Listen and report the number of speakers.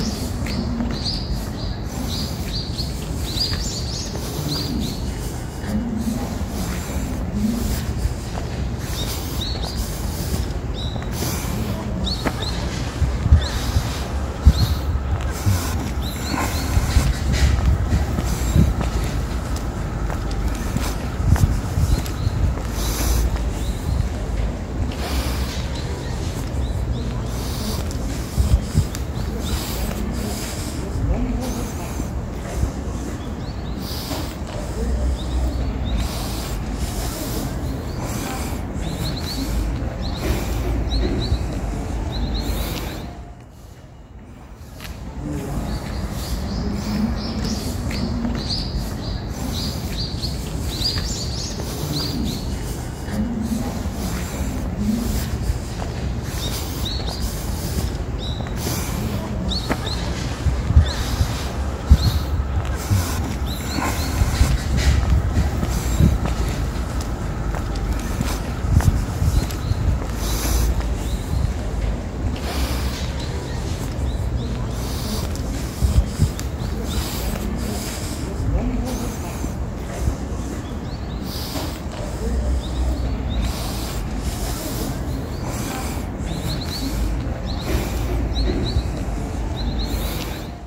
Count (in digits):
0